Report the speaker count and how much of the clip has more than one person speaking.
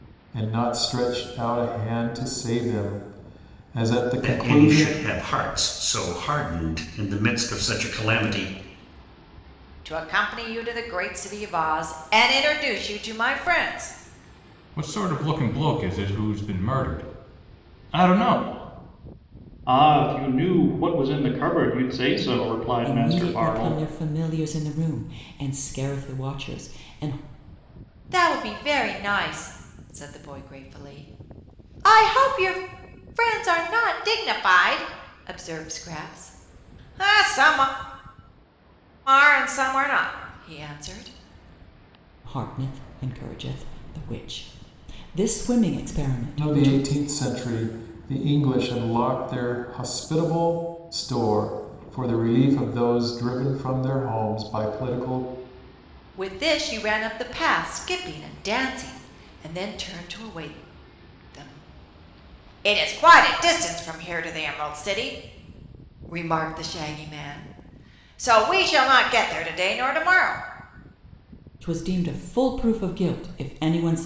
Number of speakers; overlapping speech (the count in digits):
6, about 3%